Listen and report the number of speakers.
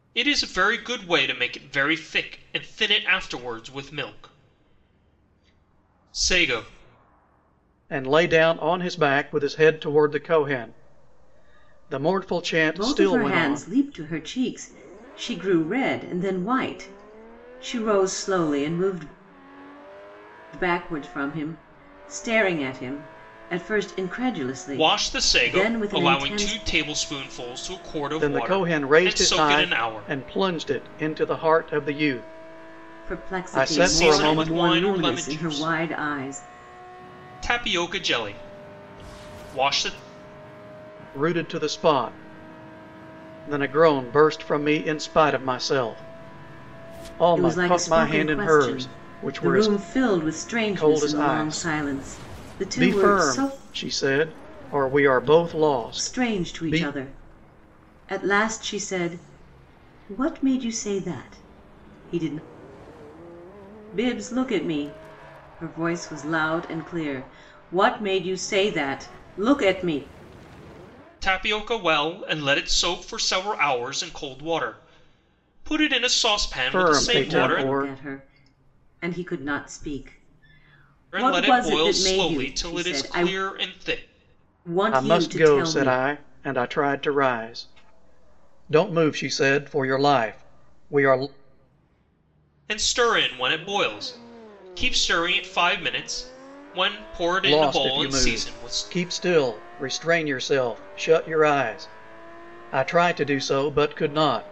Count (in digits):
3